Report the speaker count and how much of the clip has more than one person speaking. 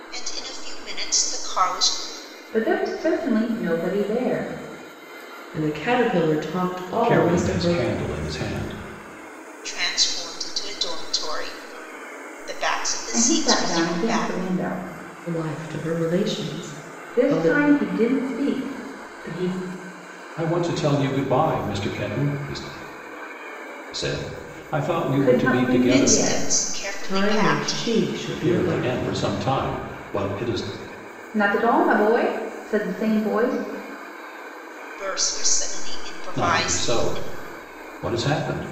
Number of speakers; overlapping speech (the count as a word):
four, about 18%